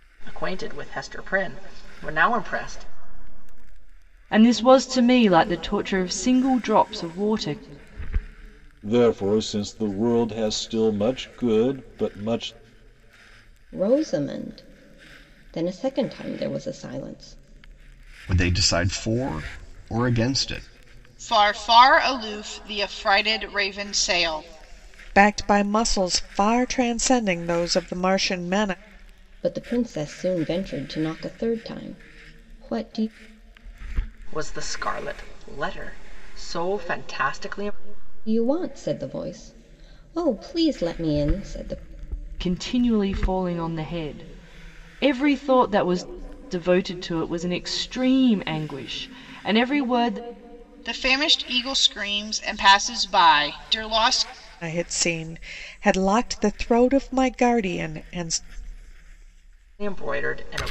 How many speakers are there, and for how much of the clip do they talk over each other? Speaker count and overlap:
7, no overlap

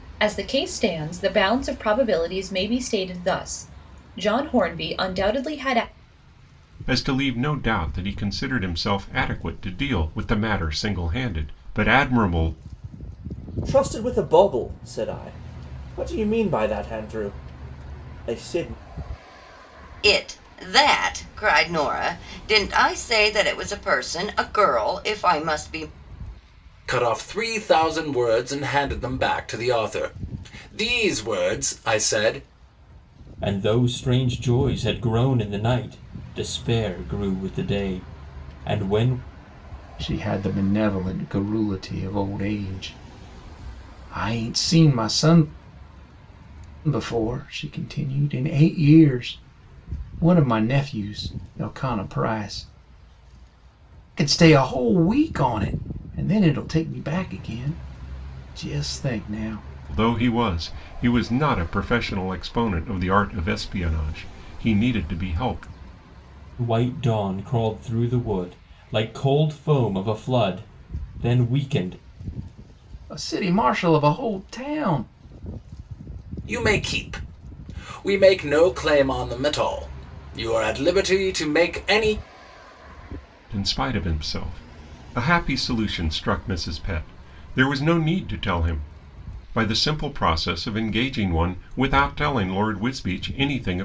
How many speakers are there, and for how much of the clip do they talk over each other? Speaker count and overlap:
7, no overlap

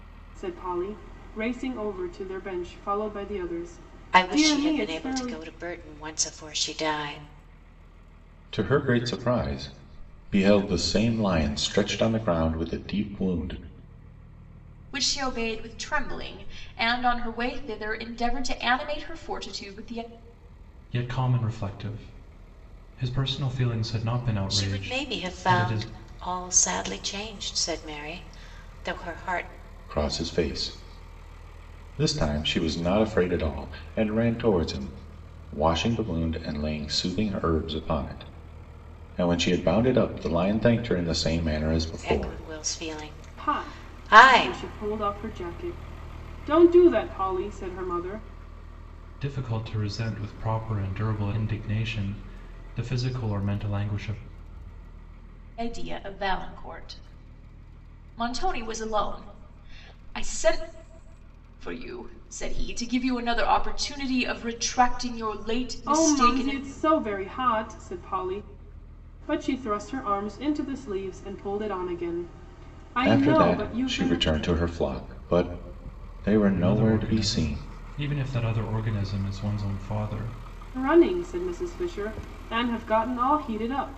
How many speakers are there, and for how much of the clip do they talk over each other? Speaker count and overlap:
5, about 9%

